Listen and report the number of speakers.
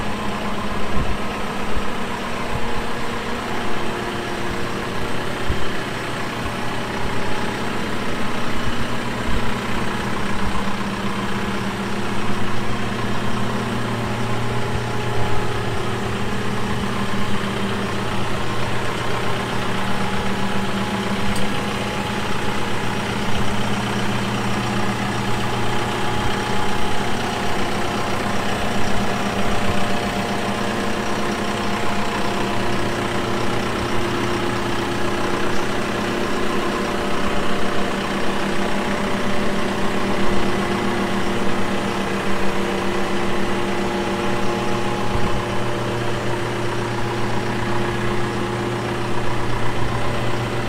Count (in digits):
0